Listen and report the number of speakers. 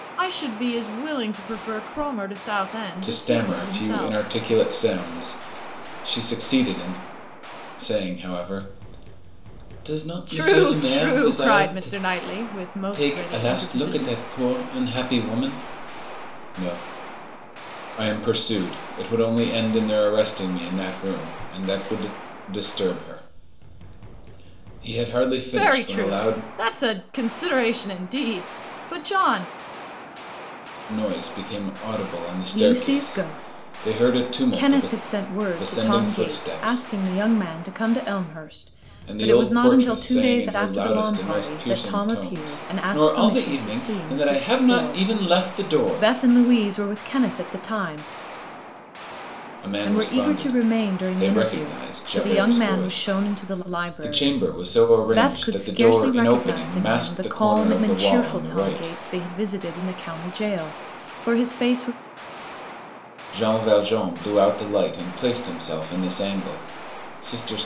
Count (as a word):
two